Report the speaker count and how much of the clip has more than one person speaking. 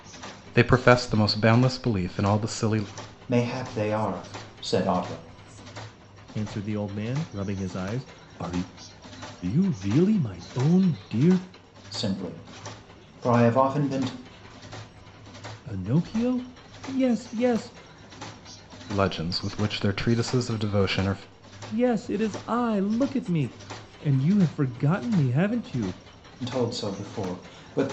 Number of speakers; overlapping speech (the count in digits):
3, no overlap